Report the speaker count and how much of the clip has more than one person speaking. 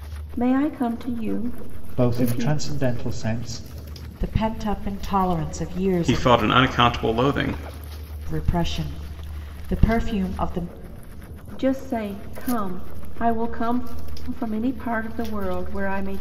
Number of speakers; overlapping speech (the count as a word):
four, about 6%